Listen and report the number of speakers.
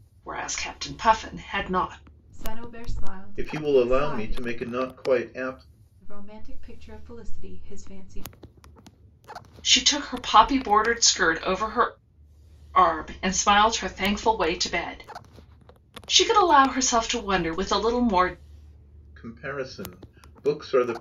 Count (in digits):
3